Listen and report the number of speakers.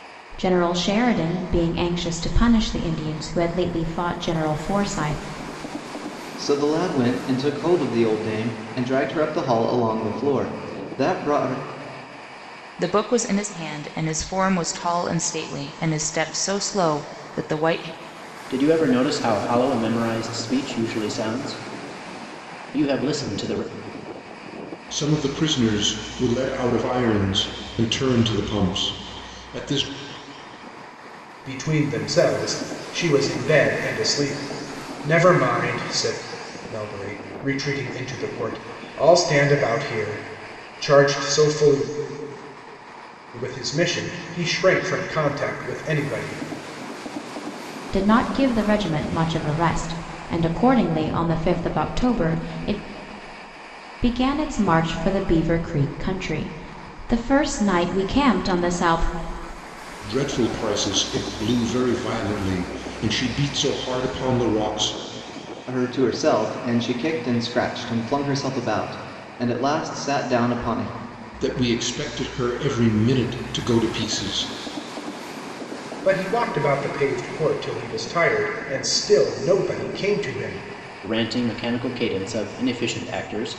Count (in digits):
6